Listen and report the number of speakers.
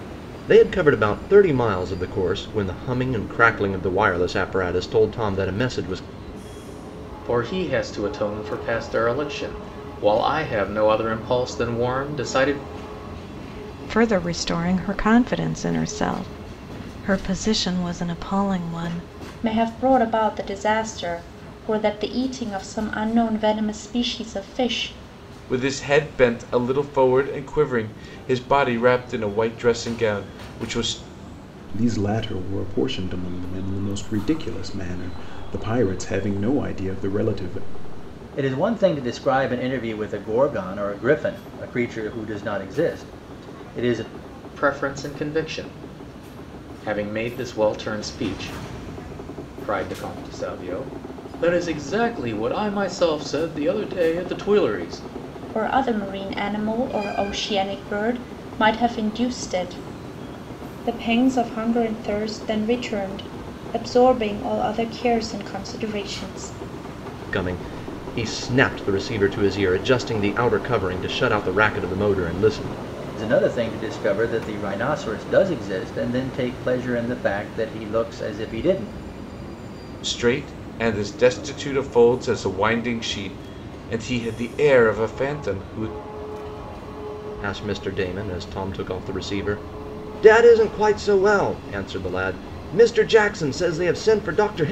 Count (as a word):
seven